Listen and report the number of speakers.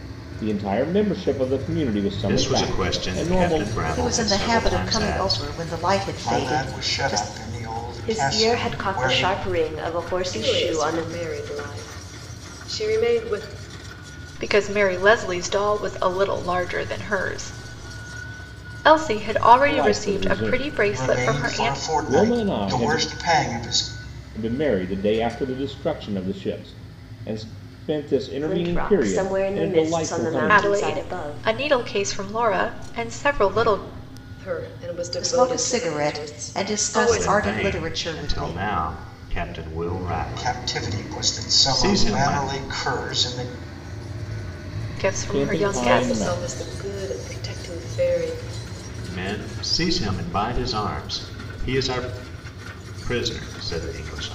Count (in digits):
7